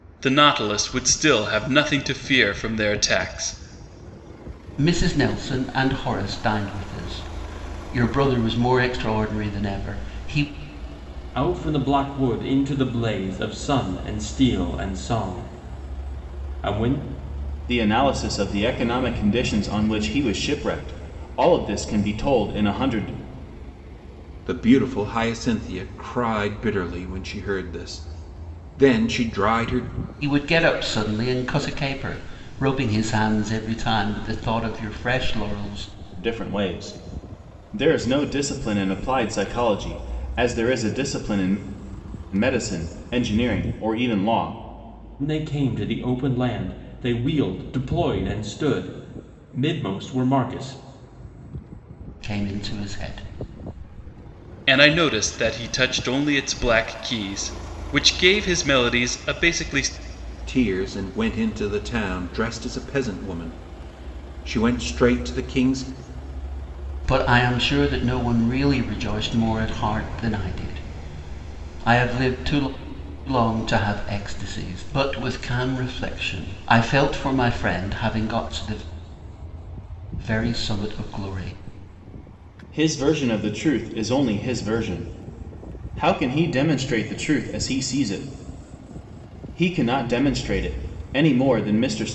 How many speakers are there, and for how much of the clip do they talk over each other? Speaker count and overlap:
five, no overlap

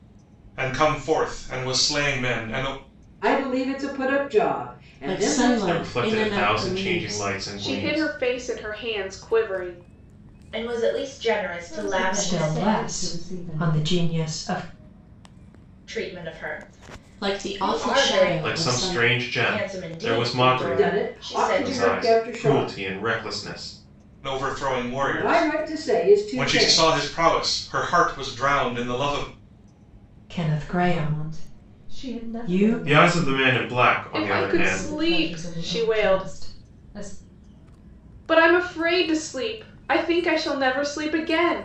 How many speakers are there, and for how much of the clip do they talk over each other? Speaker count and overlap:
eight, about 42%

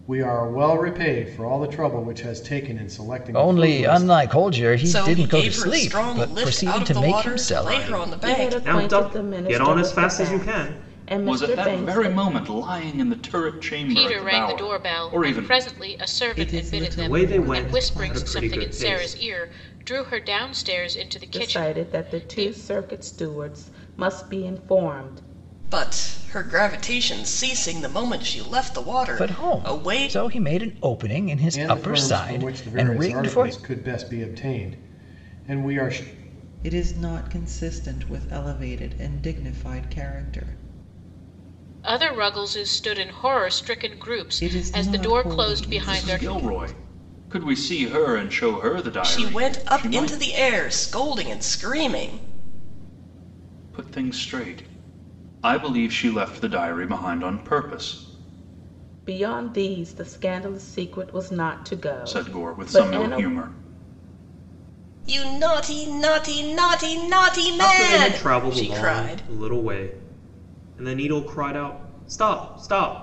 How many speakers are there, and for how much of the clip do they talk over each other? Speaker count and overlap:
eight, about 32%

